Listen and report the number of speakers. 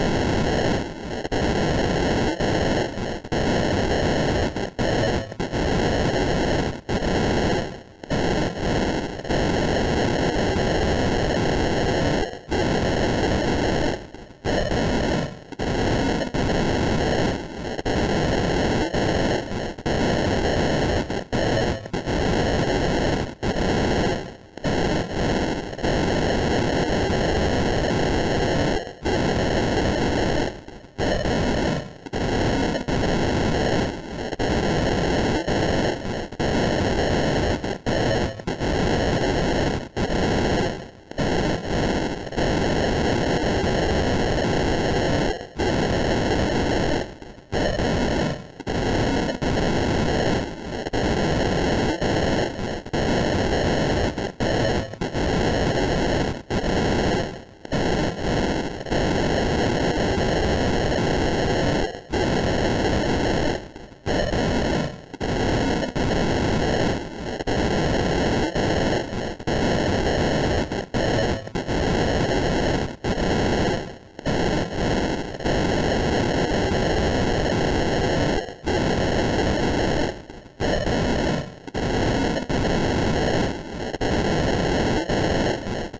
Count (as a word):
zero